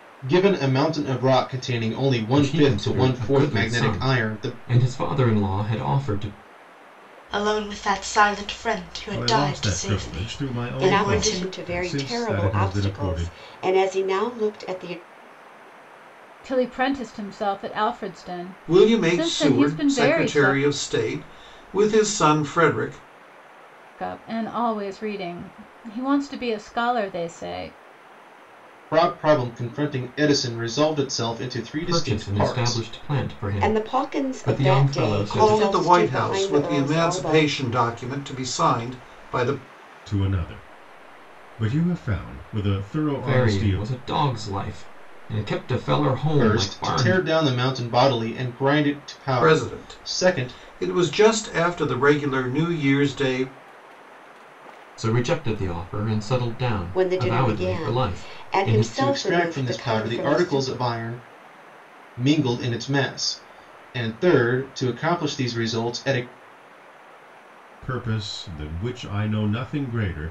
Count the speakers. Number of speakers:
seven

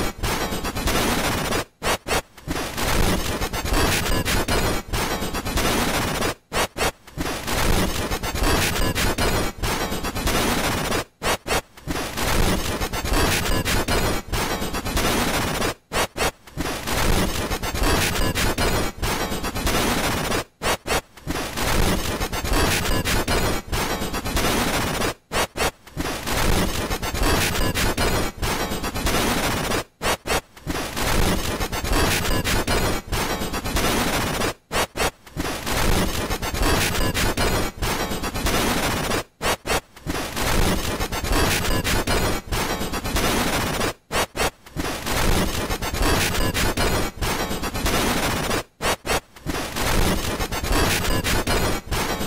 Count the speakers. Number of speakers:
zero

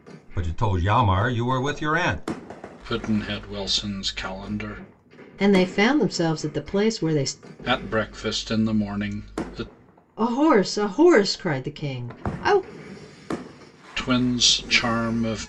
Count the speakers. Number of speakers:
three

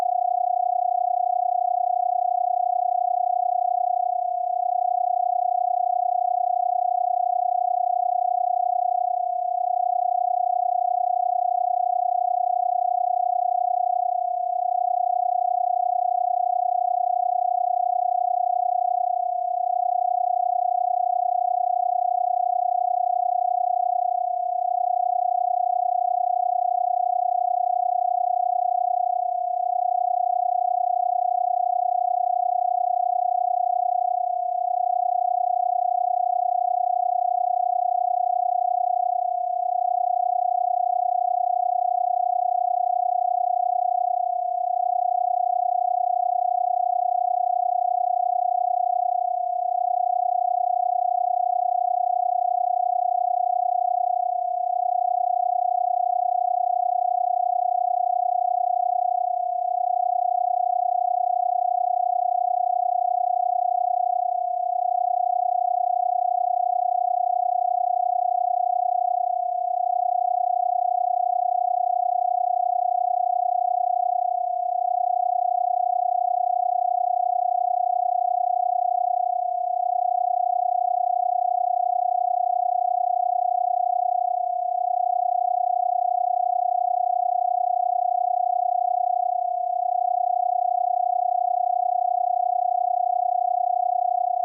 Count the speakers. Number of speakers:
zero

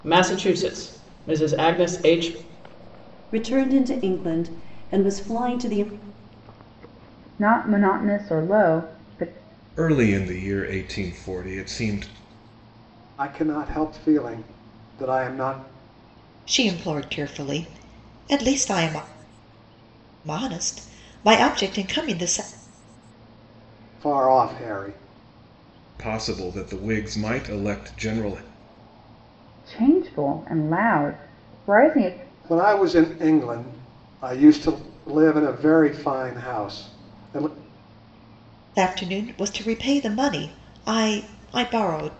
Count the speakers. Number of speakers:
six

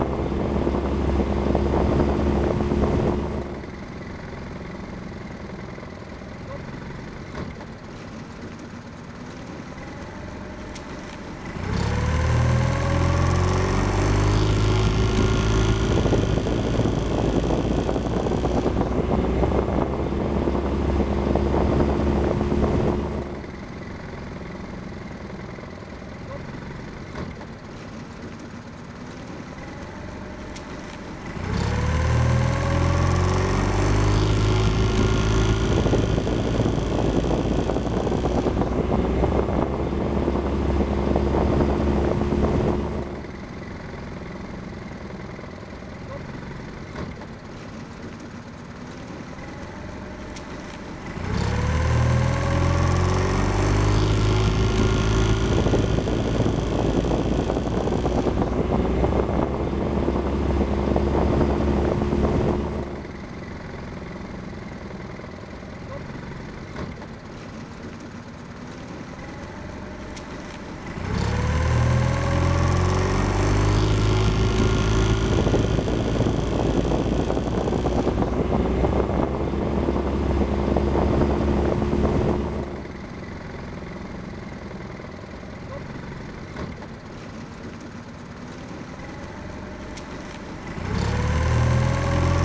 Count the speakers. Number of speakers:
zero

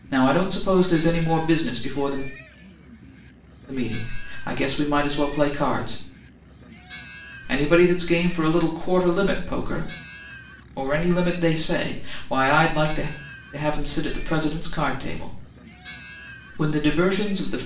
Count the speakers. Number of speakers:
one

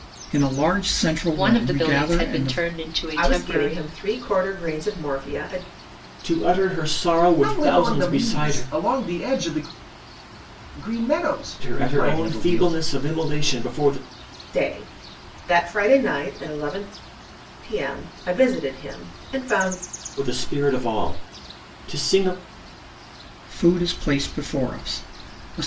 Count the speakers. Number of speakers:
five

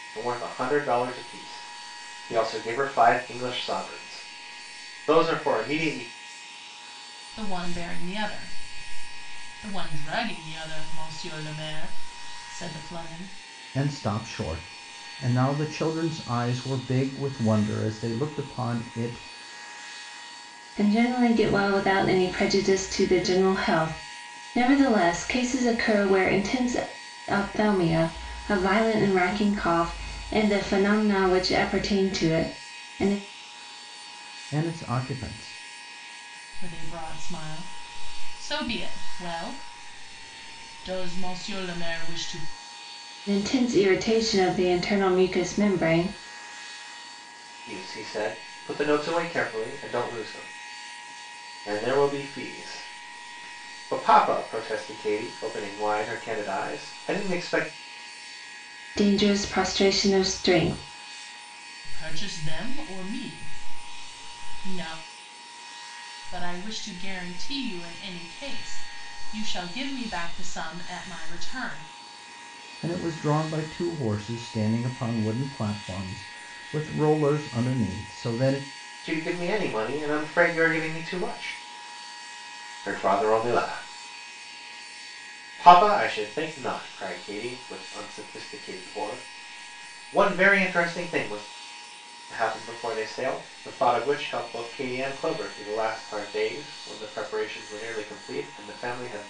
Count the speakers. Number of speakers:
four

